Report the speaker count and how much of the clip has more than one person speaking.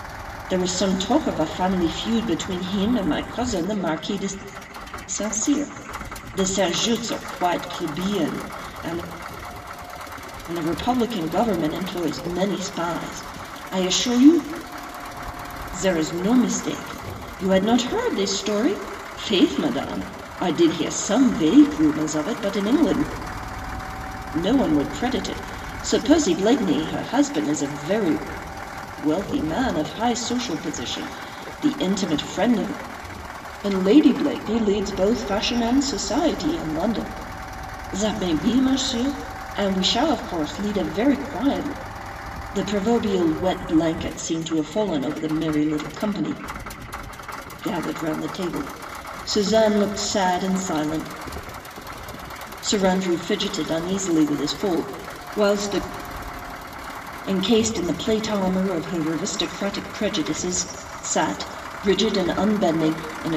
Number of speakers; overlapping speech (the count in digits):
1, no overlap